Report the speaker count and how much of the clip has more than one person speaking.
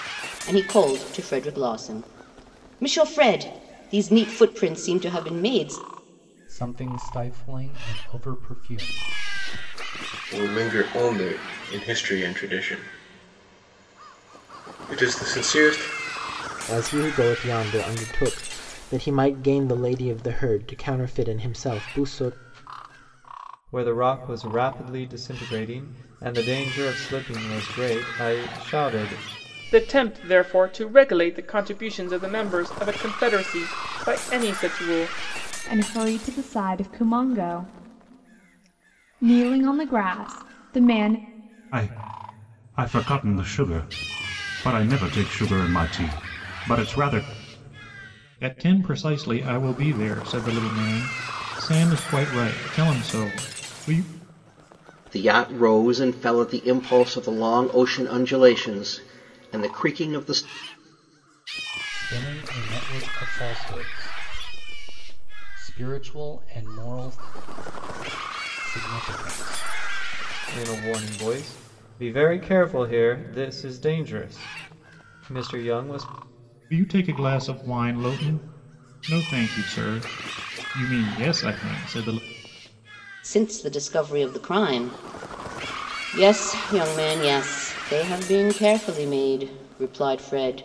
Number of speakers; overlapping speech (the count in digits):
10, no overlap